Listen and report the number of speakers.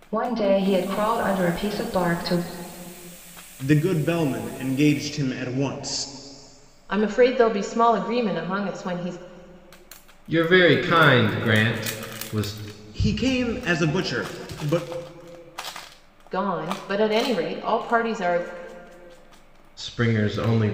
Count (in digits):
4